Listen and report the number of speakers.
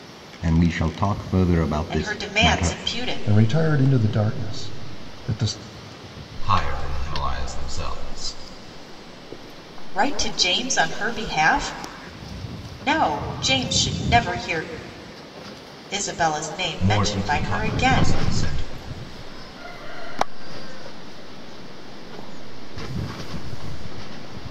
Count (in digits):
5